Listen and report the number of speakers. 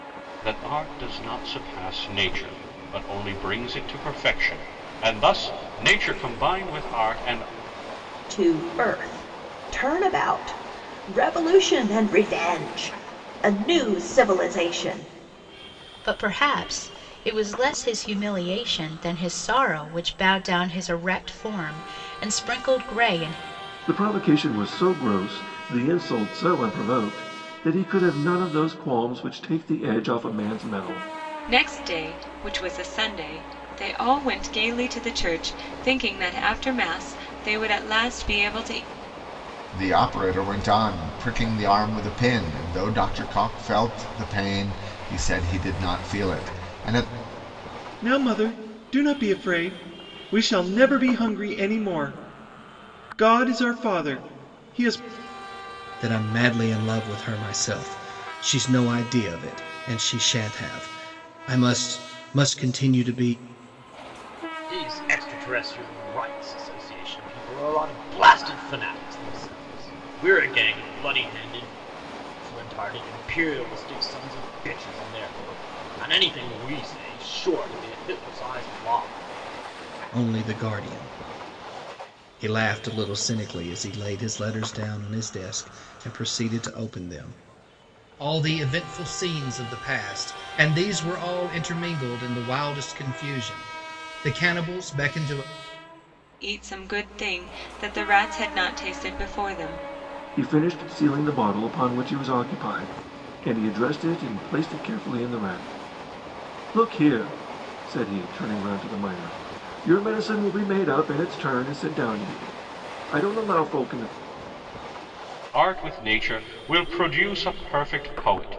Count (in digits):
9